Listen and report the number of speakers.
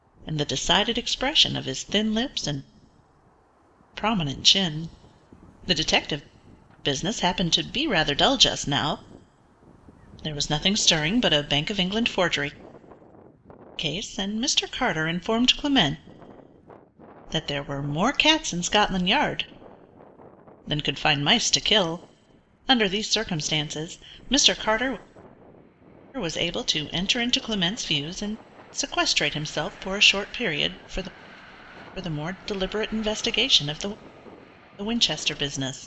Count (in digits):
1